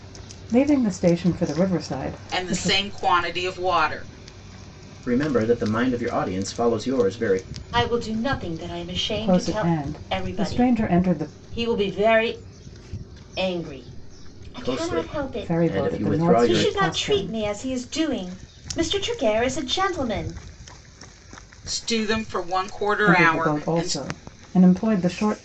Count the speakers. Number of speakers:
4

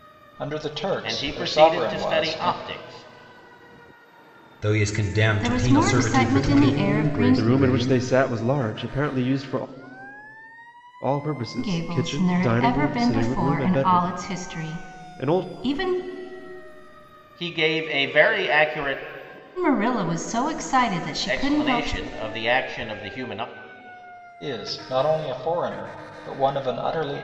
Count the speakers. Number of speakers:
6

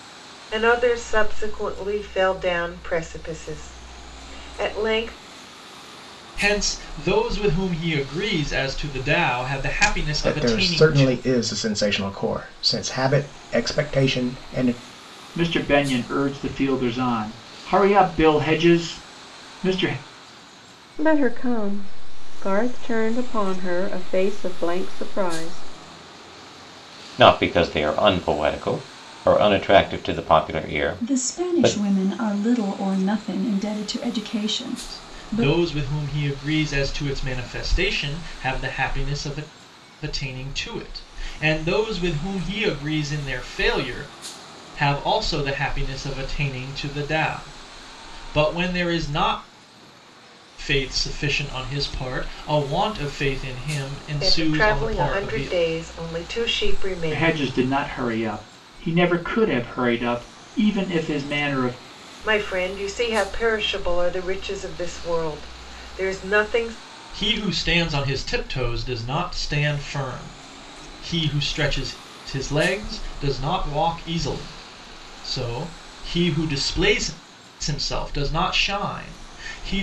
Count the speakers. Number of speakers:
7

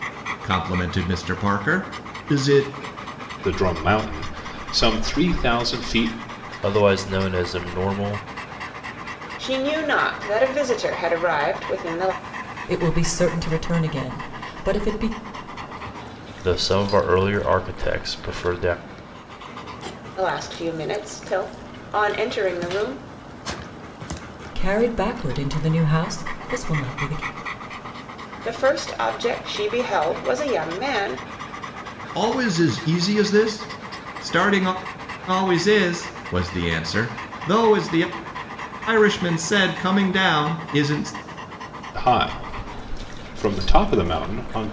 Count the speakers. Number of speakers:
5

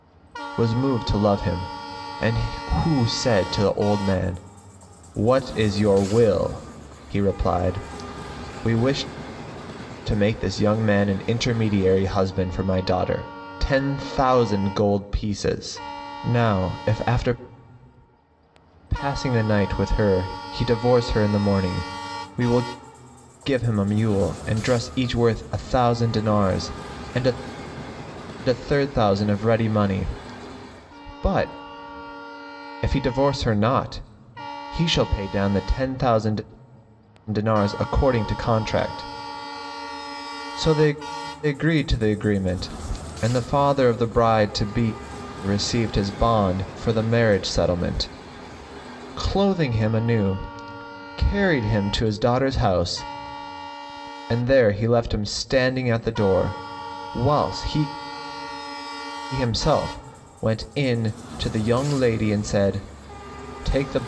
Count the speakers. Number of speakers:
1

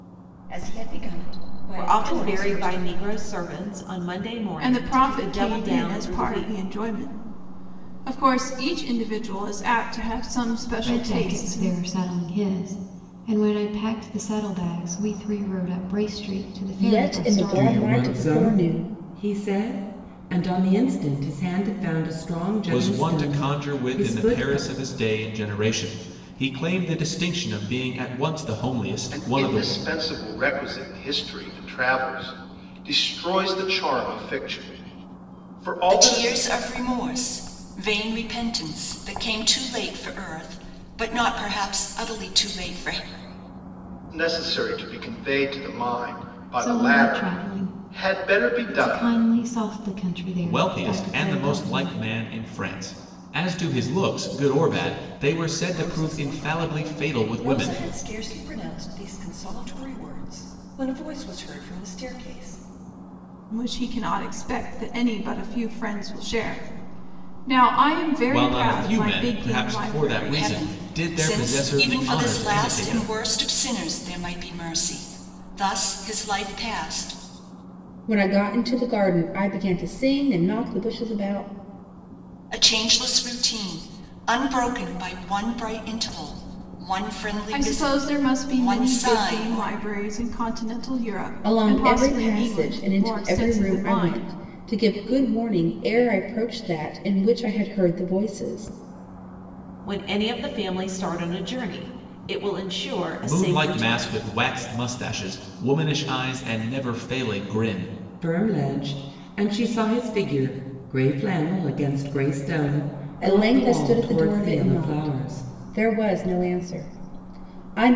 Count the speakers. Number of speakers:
9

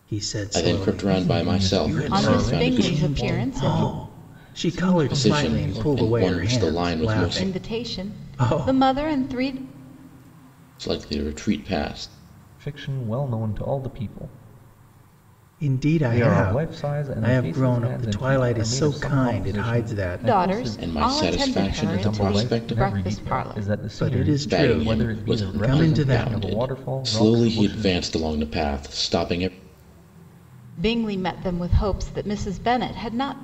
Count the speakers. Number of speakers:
4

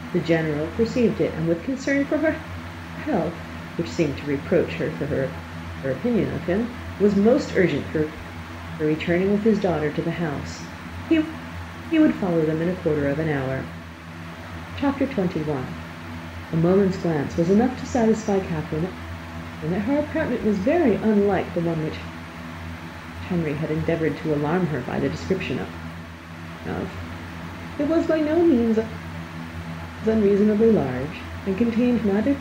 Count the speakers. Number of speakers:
1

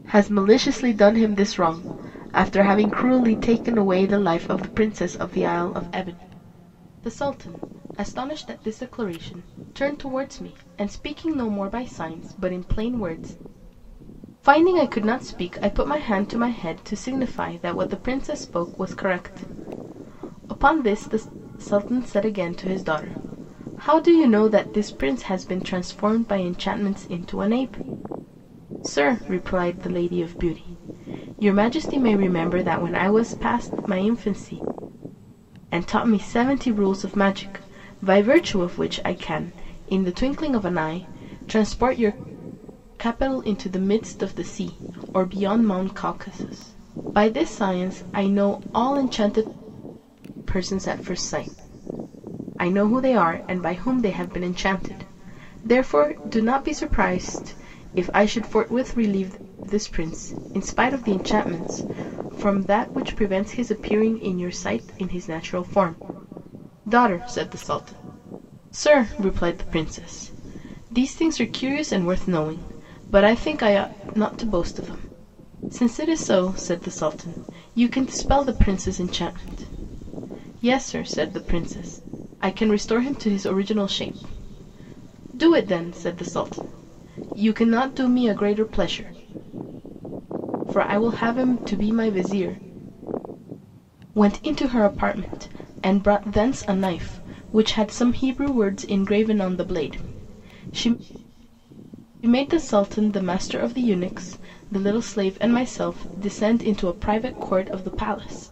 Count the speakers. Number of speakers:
1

